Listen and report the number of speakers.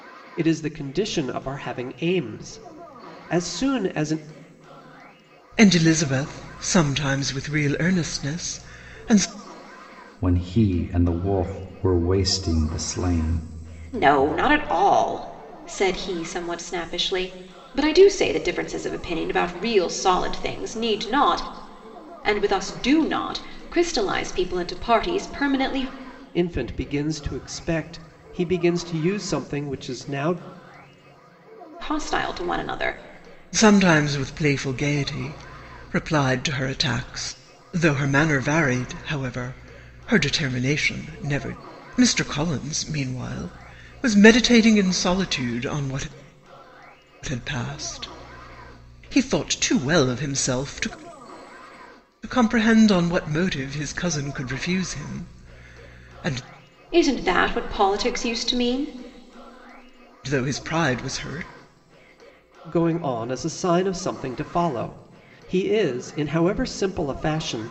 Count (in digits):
4